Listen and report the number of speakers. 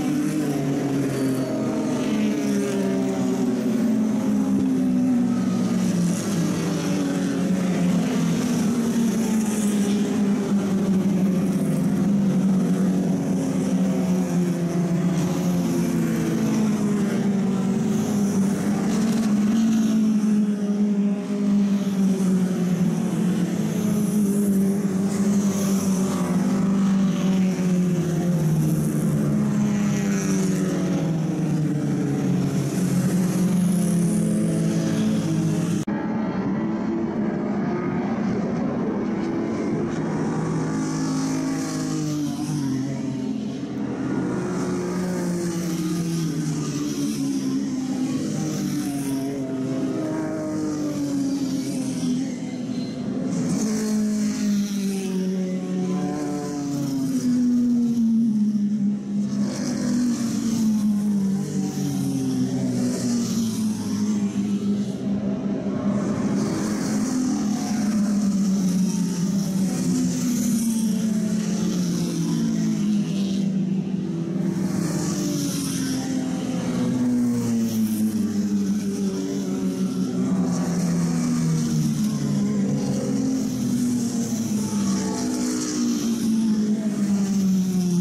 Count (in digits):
0